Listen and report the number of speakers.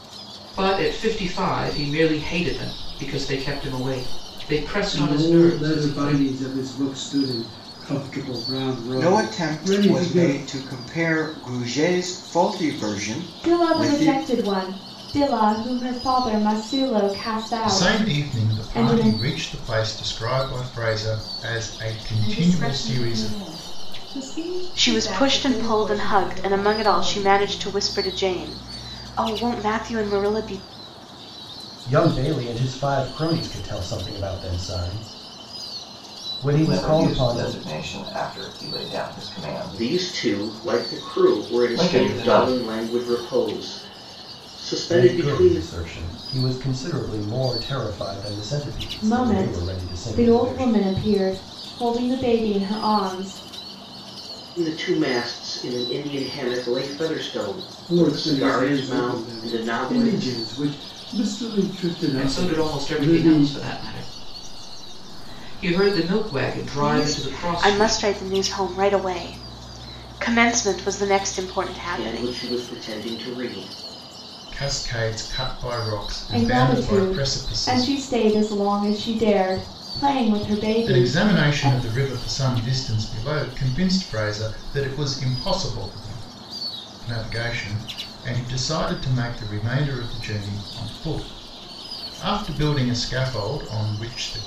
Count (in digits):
10